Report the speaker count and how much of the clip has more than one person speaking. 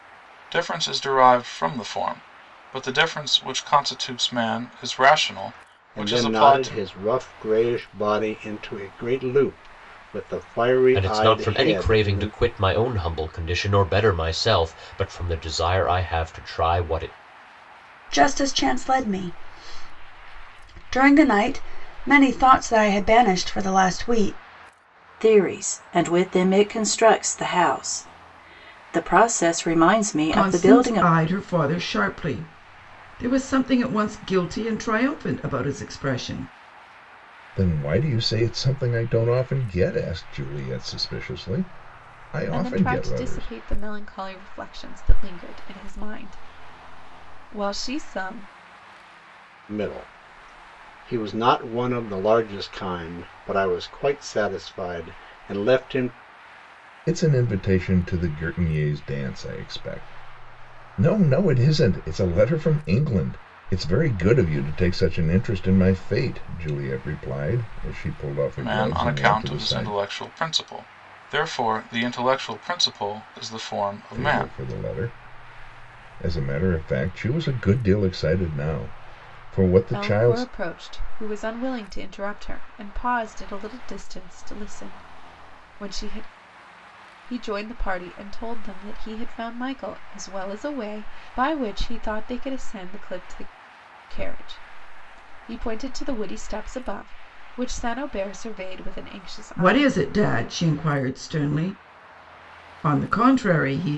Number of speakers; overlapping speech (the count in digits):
8, about 8%